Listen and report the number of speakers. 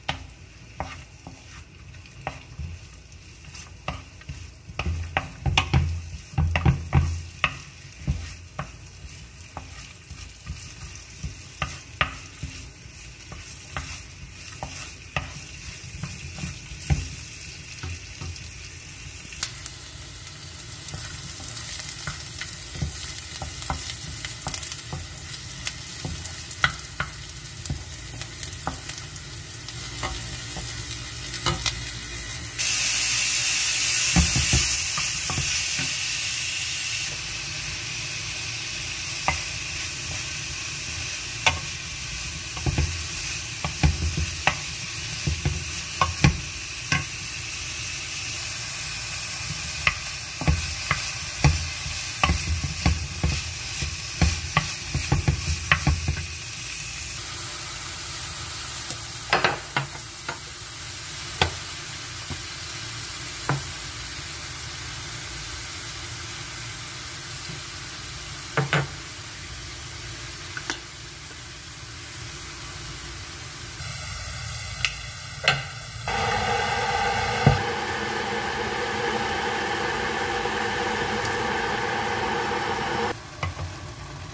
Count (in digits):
0